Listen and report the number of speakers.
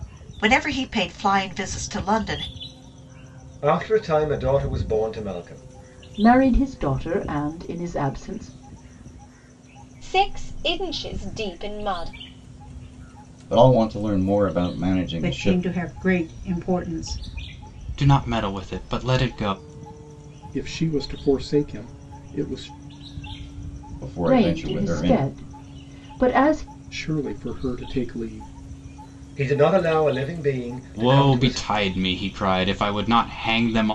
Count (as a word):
eight